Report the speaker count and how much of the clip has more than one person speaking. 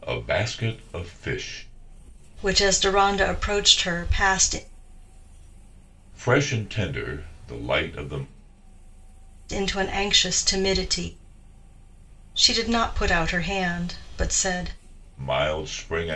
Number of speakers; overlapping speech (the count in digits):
2, no overlap